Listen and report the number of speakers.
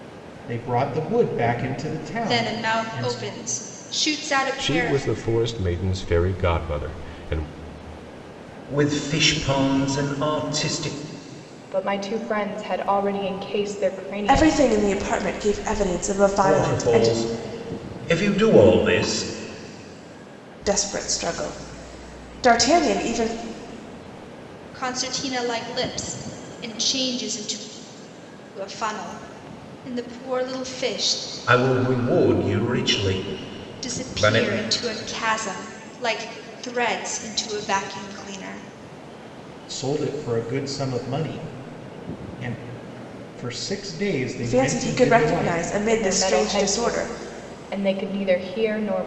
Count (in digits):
6